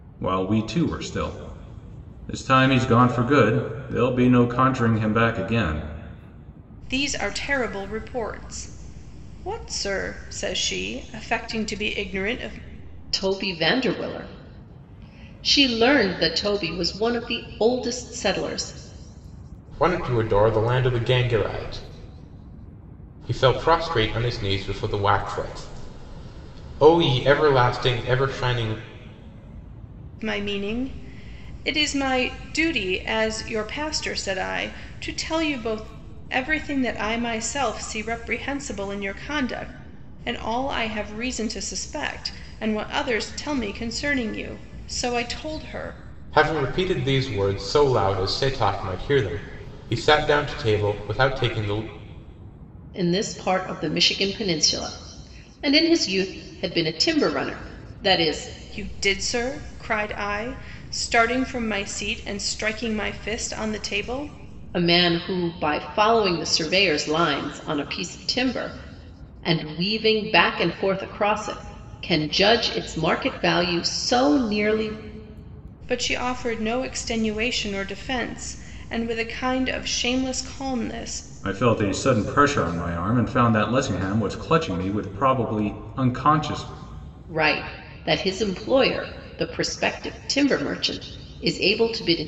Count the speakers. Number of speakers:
4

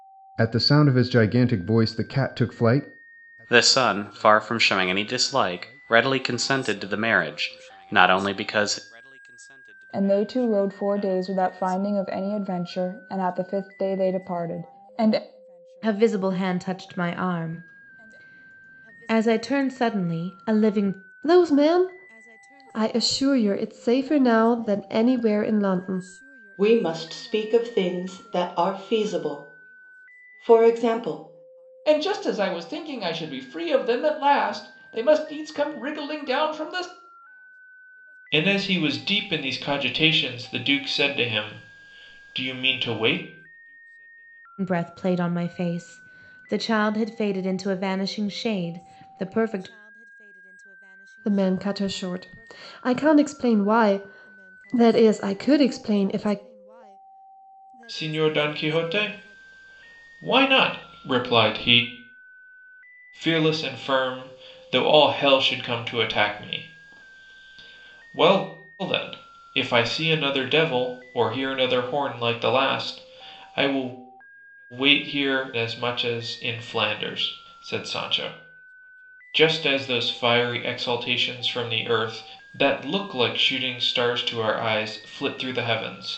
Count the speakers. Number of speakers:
8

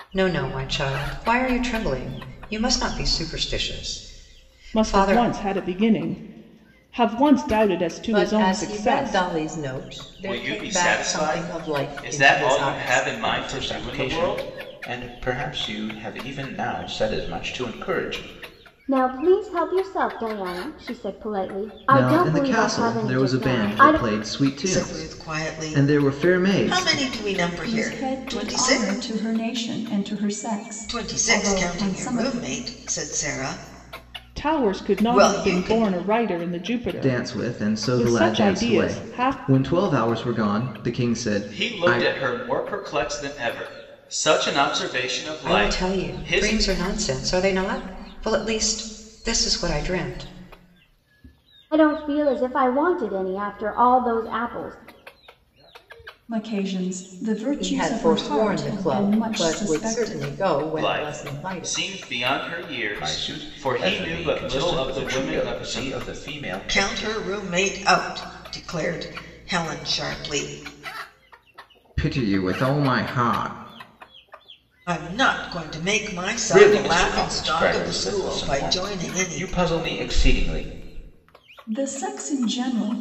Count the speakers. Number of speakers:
9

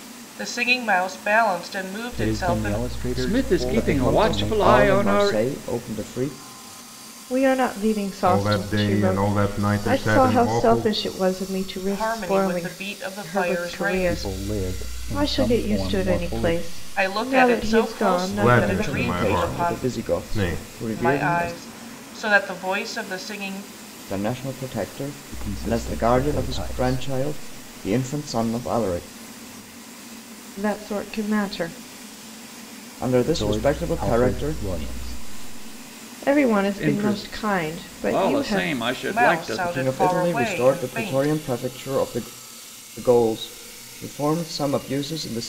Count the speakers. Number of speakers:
6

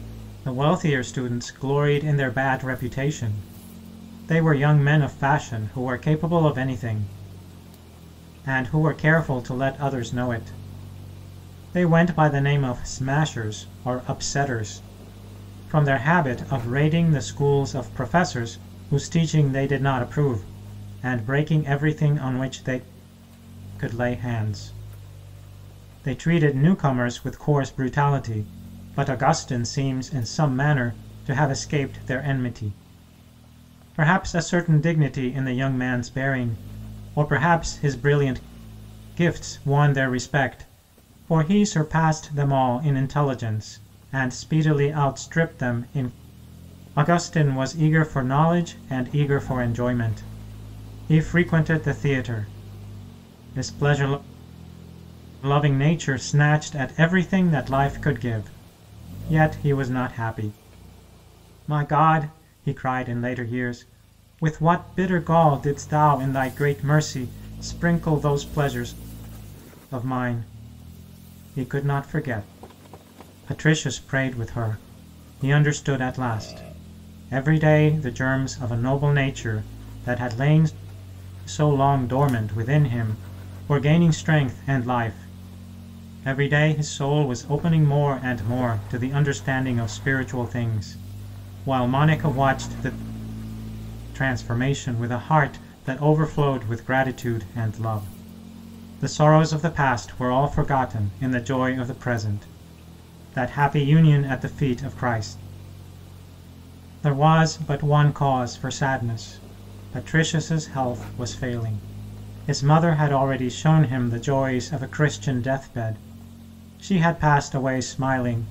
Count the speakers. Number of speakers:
1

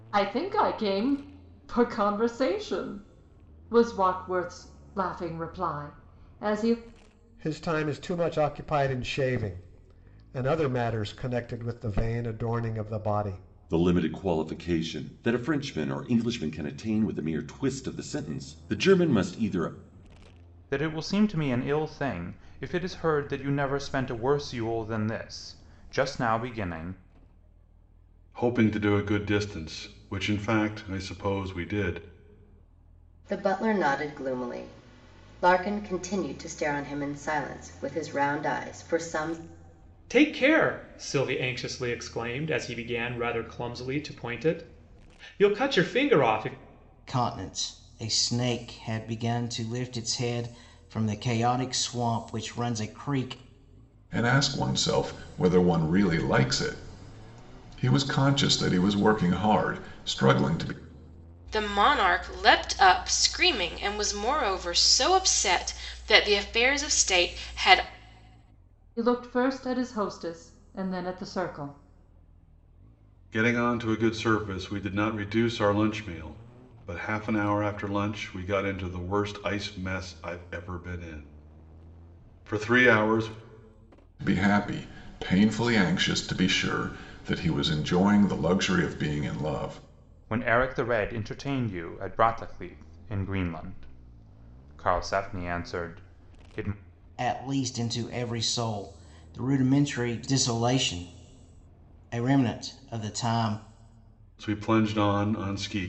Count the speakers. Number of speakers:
10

